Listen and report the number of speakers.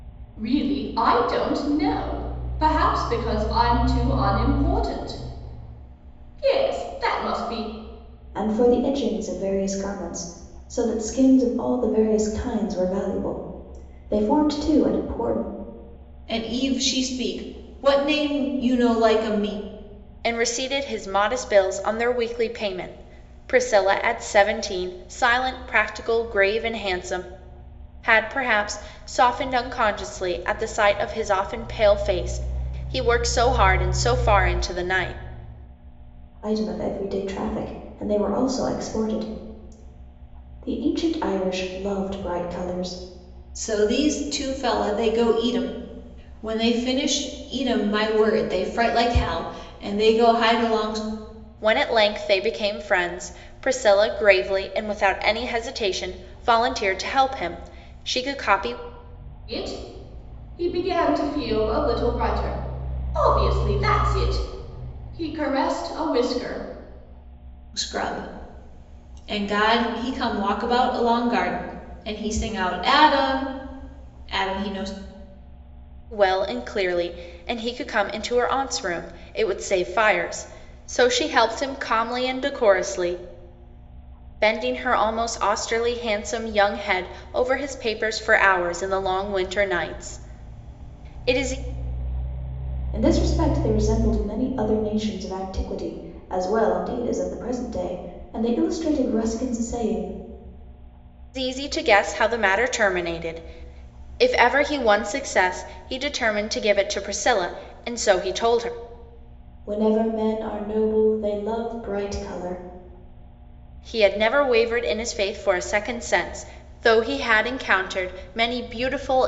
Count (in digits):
4